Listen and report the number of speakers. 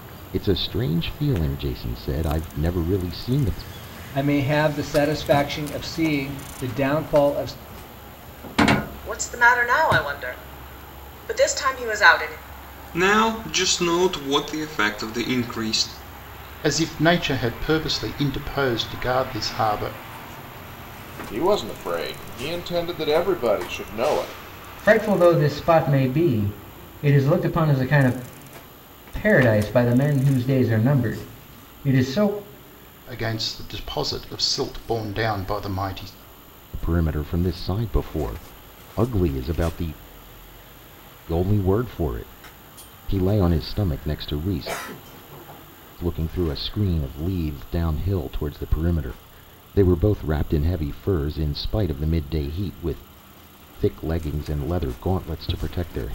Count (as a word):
seven